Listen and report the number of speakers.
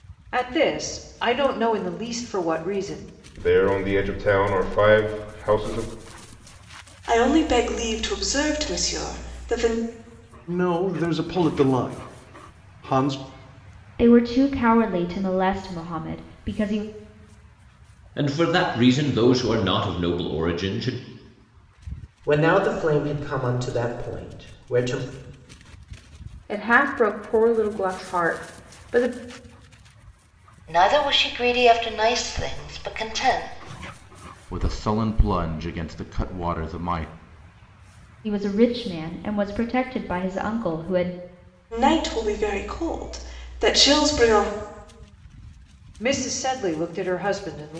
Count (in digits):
10